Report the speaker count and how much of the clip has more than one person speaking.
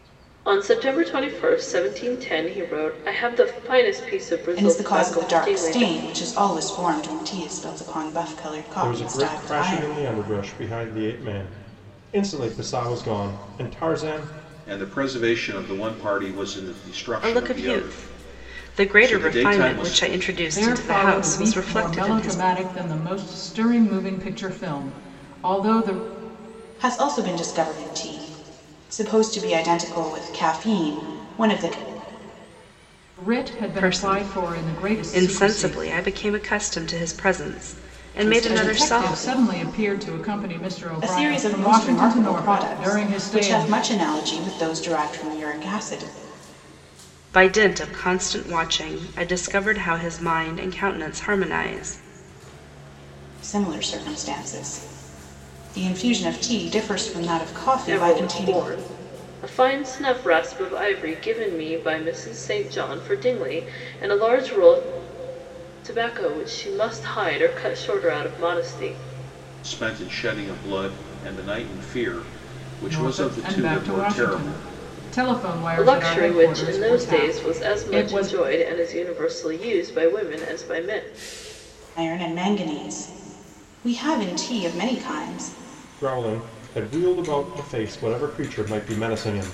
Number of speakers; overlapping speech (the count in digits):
6, about 21%